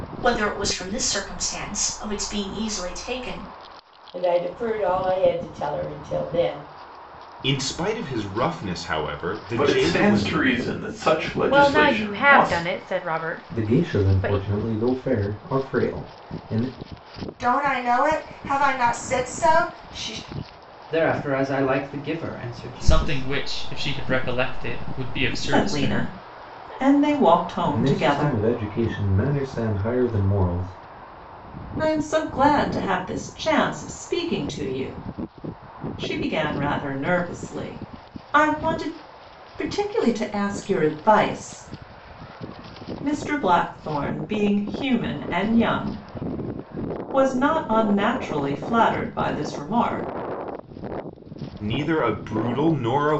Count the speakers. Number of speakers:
ten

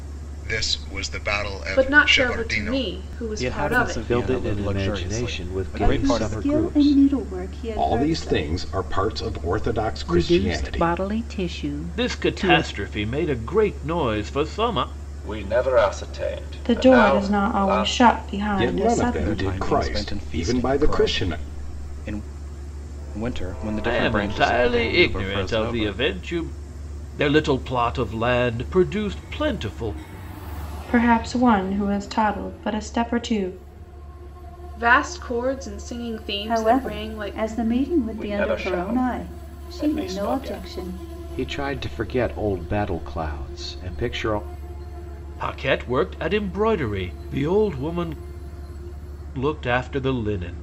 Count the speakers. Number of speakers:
ten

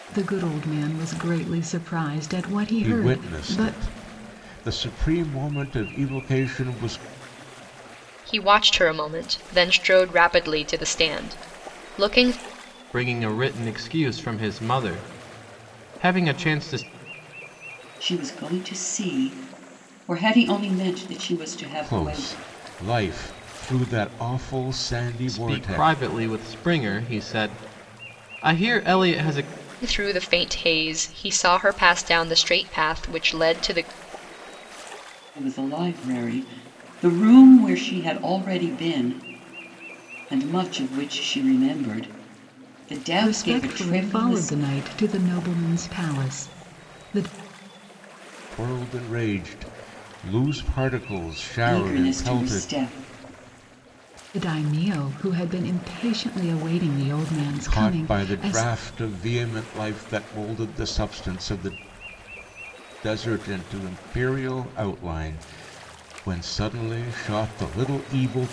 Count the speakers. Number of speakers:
five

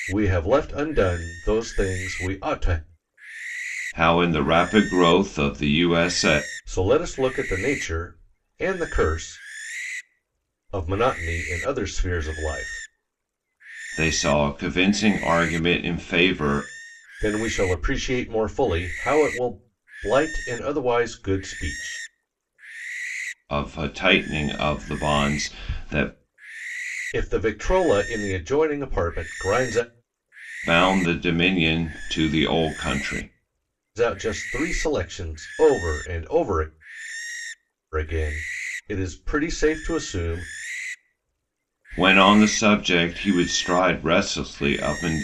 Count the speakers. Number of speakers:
two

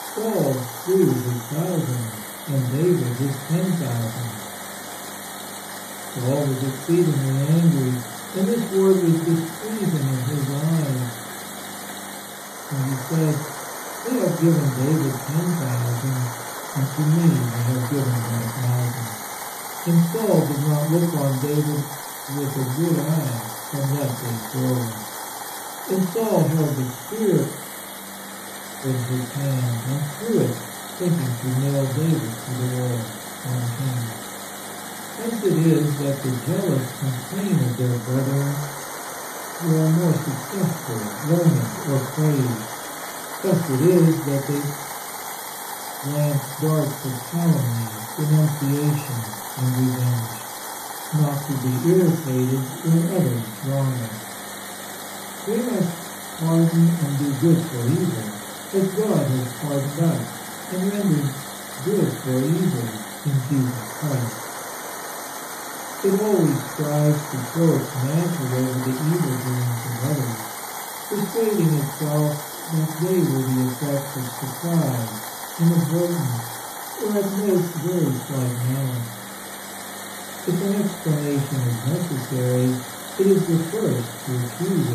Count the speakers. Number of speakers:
one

